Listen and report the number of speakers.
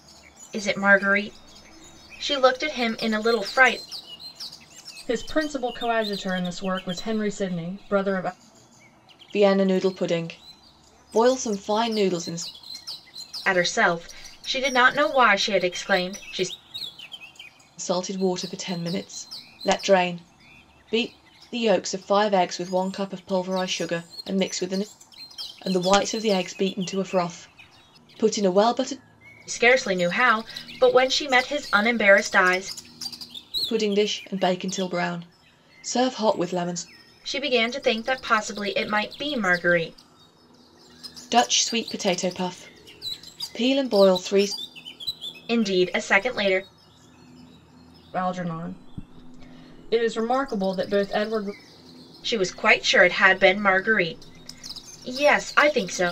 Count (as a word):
three